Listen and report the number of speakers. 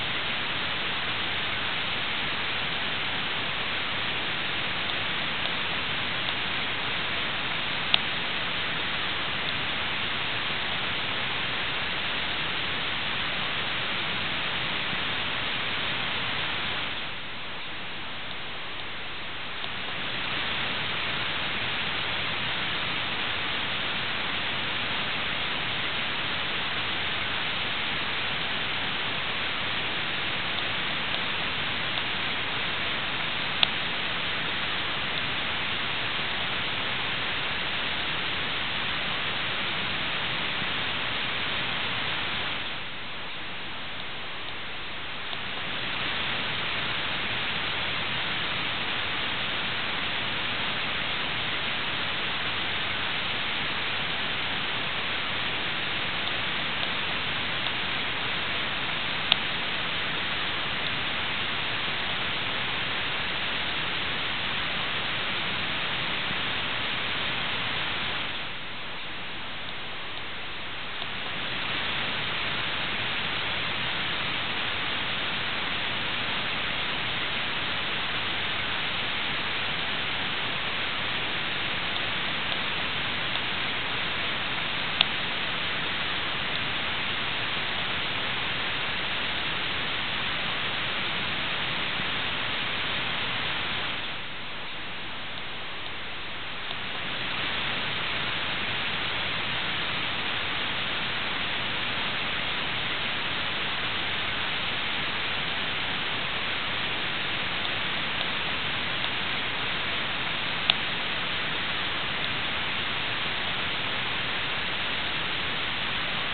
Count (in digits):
0